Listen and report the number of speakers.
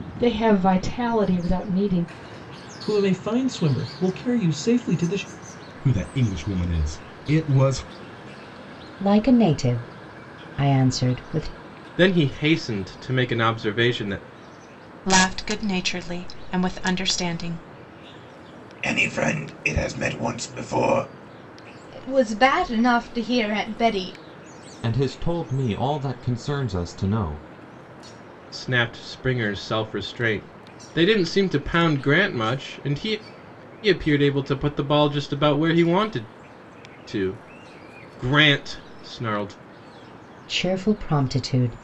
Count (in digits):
9